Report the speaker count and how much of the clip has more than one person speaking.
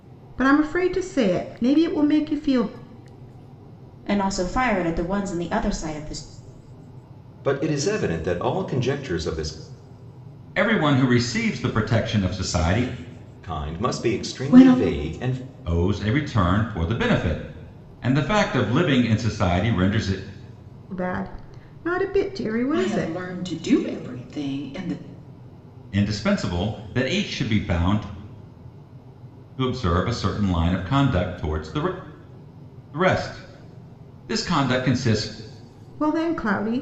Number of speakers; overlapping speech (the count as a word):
five, about 6%